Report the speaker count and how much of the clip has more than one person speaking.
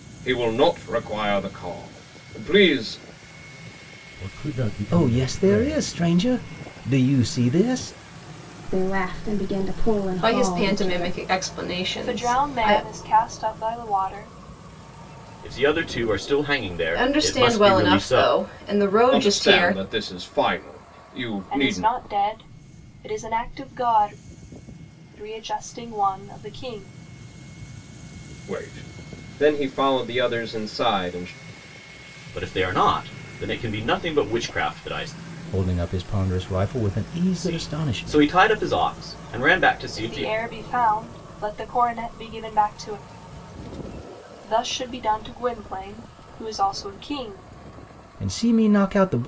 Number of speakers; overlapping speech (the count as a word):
seven, about 14%